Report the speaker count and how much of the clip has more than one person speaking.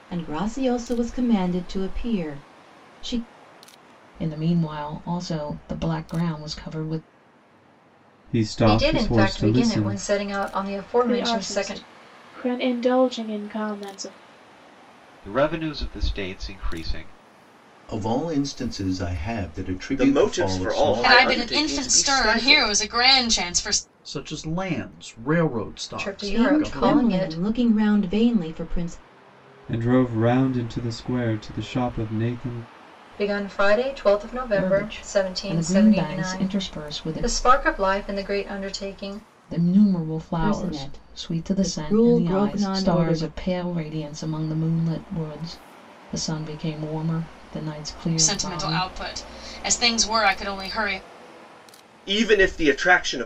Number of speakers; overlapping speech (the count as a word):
ten, about 24%